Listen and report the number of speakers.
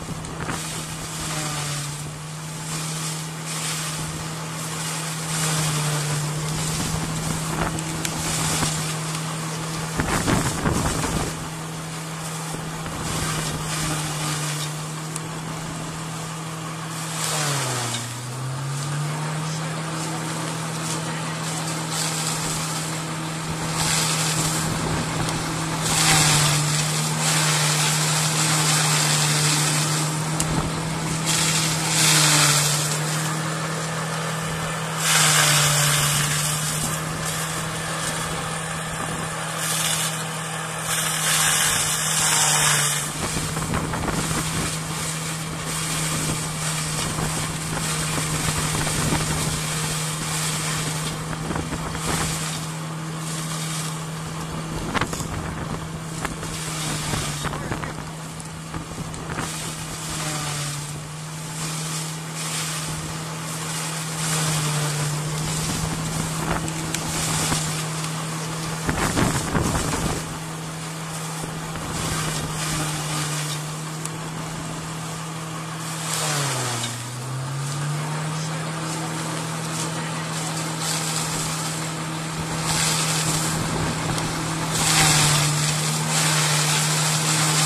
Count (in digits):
0